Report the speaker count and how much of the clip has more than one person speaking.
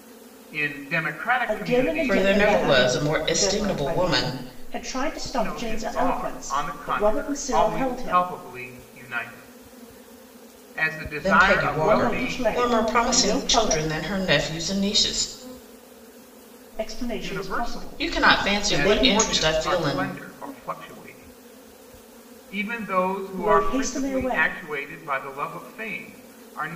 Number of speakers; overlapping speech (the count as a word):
three, about 47%